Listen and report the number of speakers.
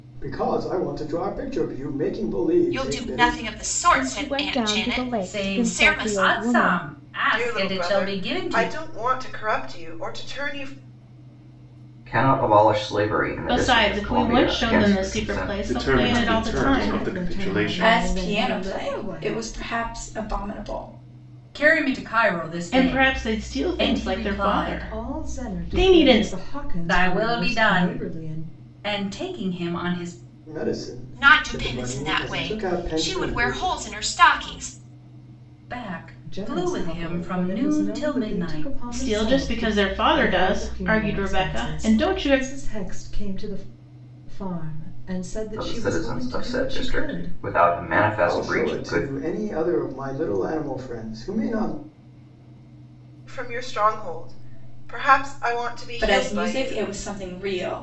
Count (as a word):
ten